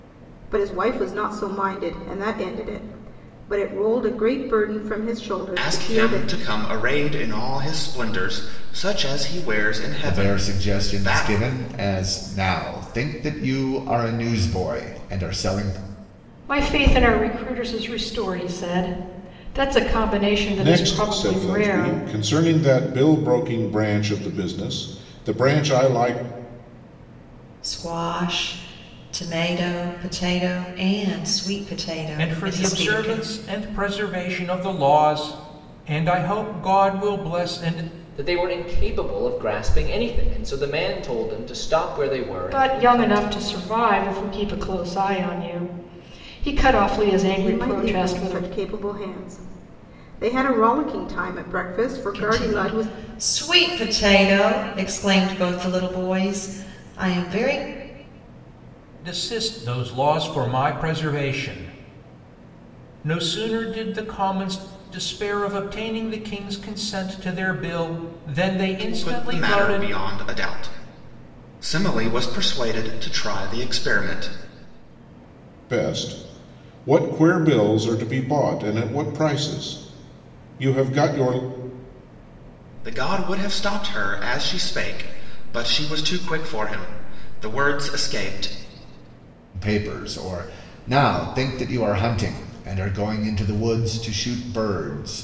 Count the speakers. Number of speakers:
8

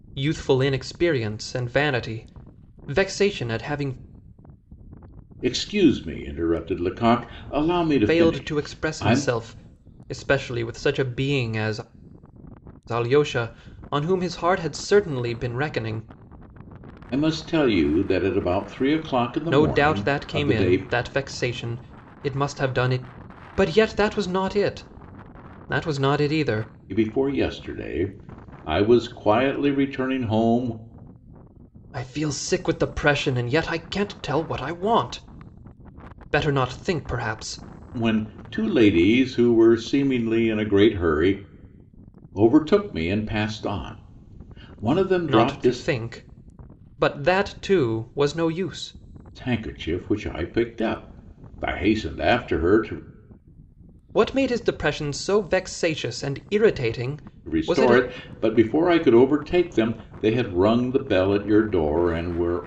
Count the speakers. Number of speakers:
2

